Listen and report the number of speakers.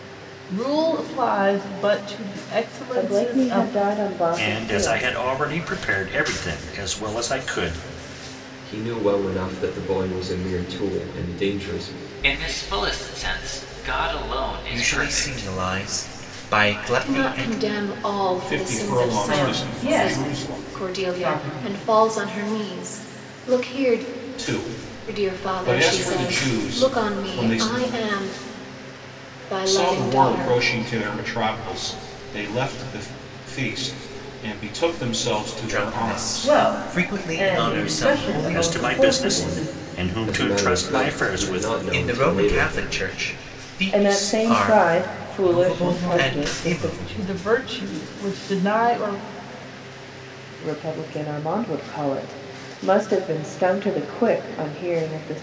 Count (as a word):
nine